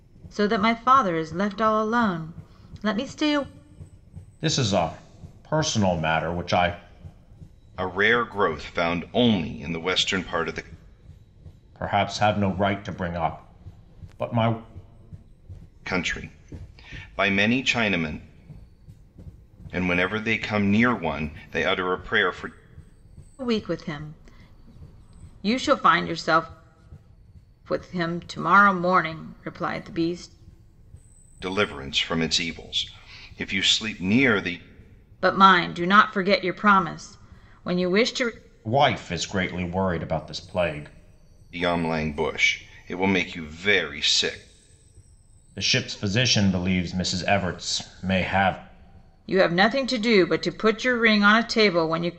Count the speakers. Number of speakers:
three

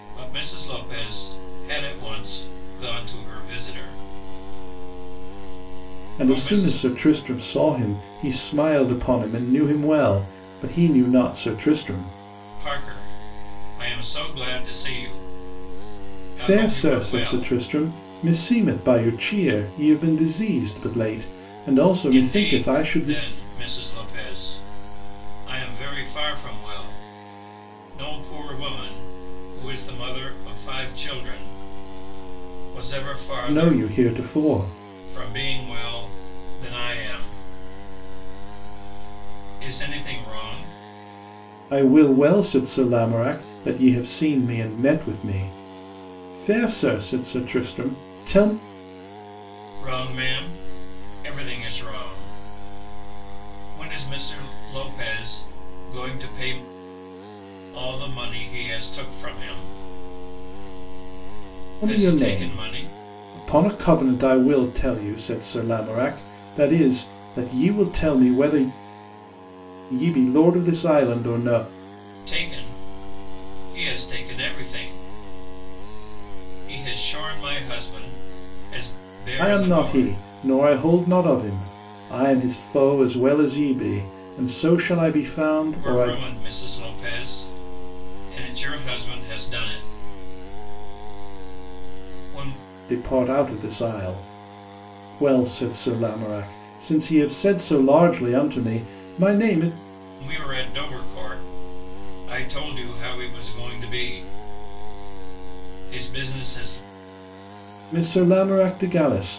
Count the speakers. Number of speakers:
two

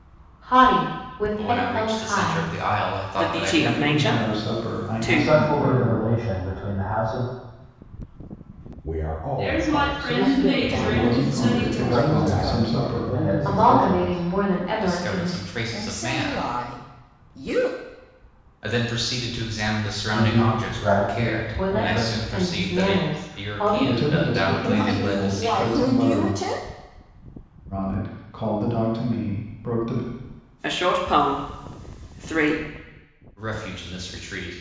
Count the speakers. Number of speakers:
eight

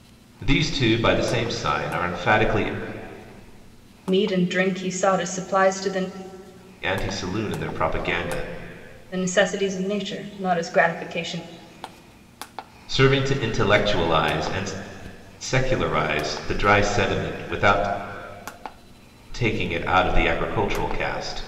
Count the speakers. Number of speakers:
two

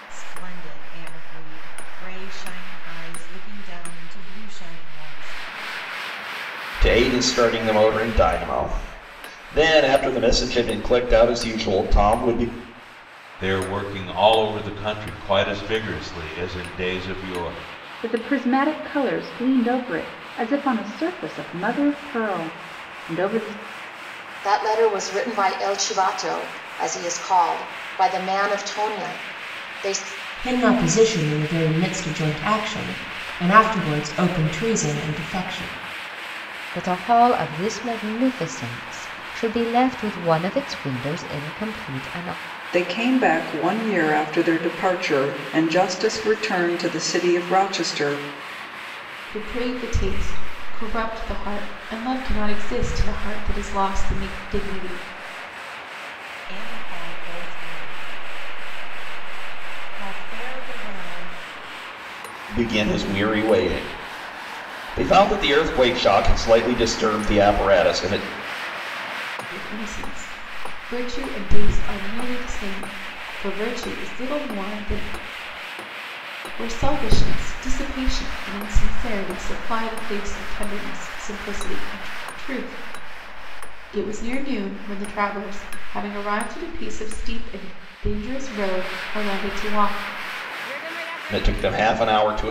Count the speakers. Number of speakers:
nine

